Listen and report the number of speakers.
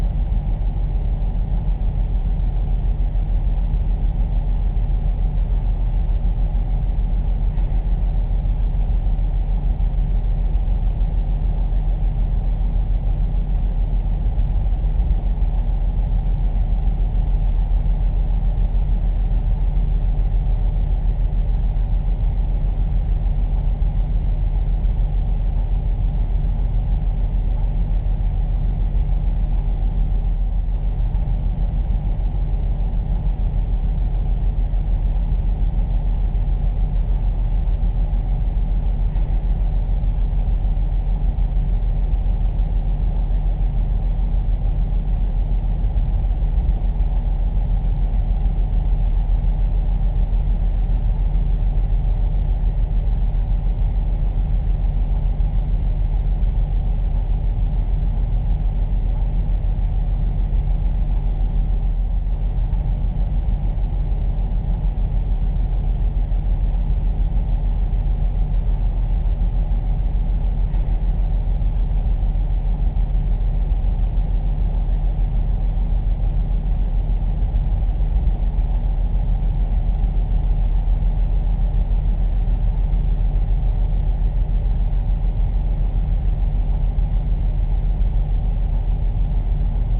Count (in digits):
0